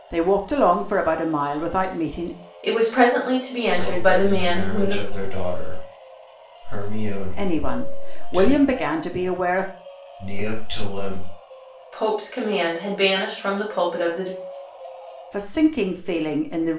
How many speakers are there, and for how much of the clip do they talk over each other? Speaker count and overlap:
3, about 16%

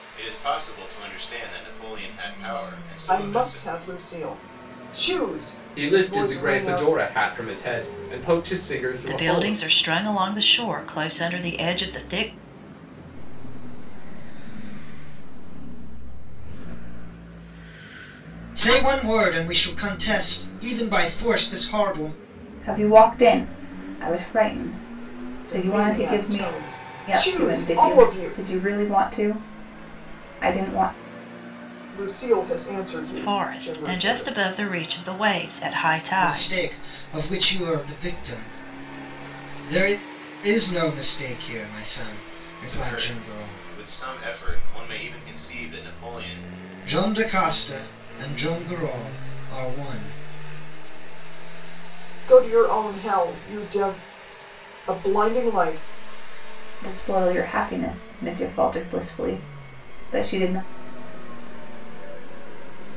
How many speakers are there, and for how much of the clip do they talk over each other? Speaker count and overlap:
7, about 18%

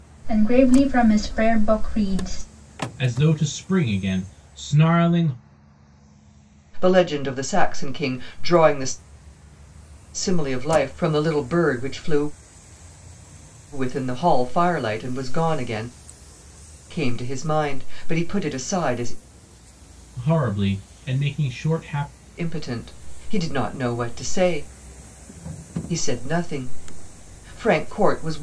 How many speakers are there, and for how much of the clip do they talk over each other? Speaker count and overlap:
3, no overlap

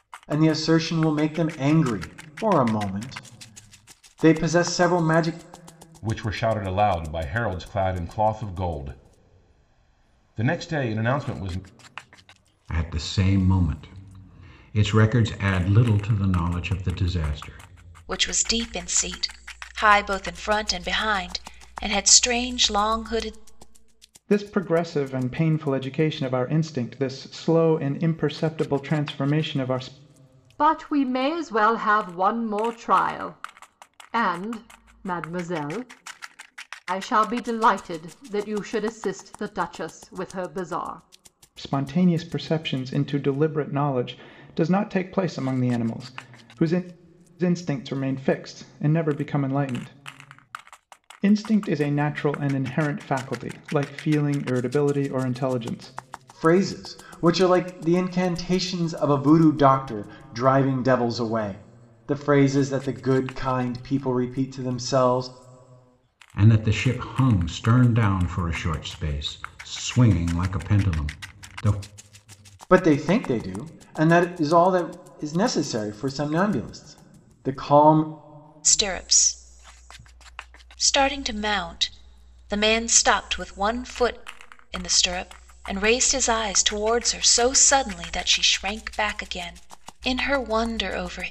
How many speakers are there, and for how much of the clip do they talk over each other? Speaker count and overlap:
6, no overlap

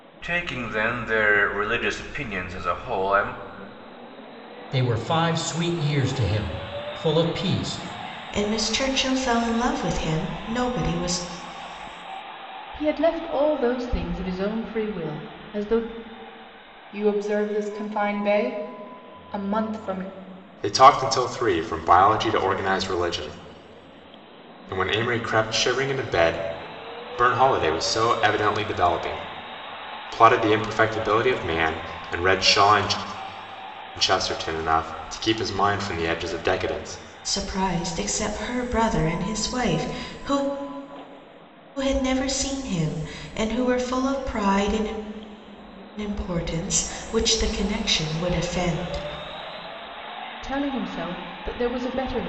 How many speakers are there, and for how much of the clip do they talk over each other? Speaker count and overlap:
6, no overlap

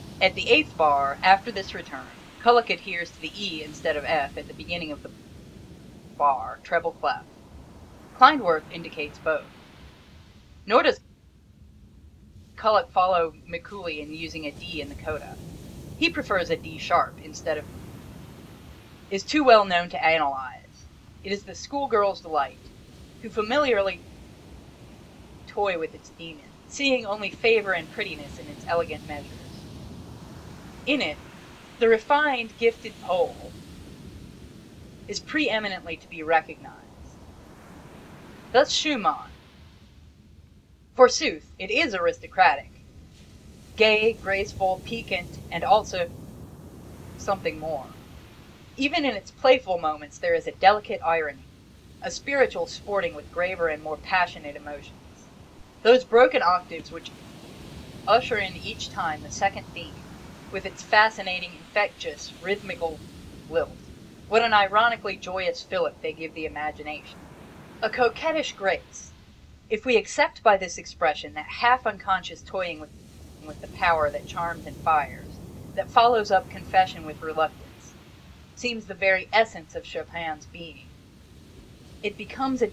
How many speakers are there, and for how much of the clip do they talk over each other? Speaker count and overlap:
1, no overlap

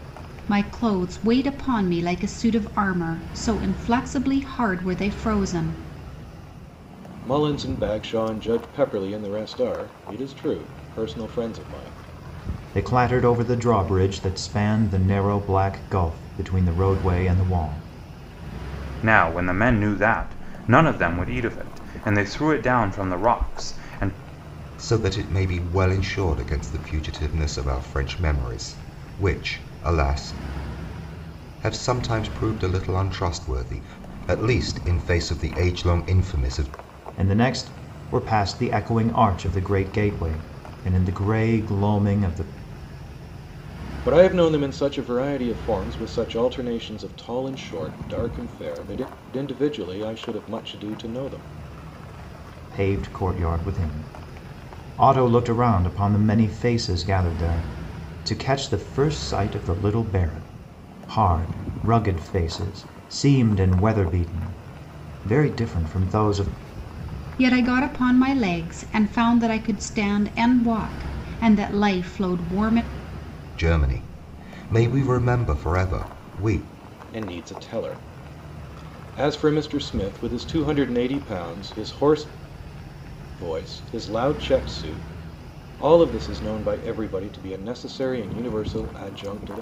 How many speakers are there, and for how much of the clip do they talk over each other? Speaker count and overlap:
5, no overlap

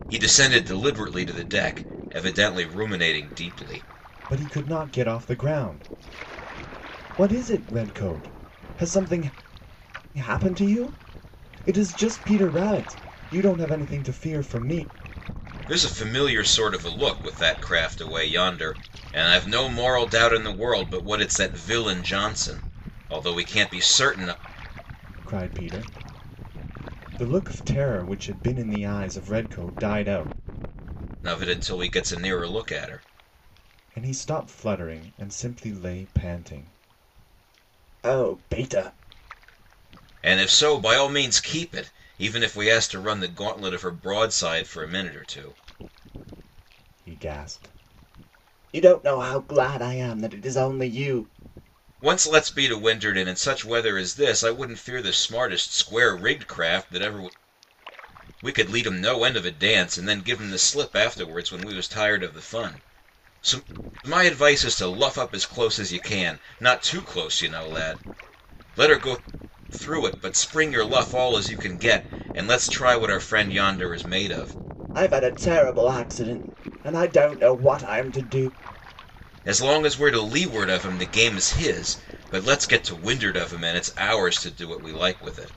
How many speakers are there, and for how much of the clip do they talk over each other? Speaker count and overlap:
2, no overlap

